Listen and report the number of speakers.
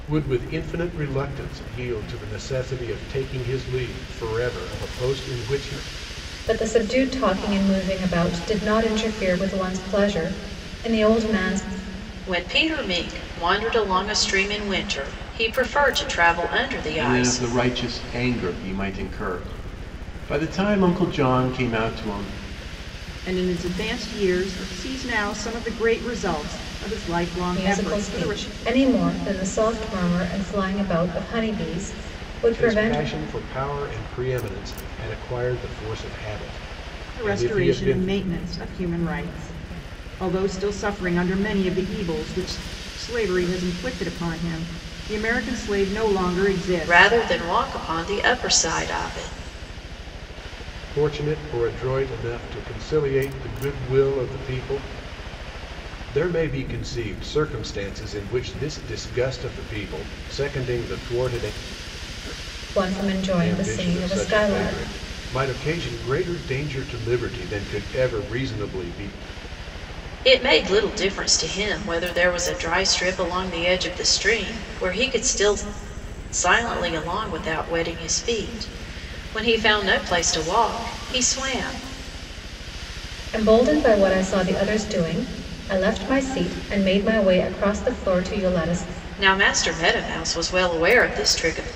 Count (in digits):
5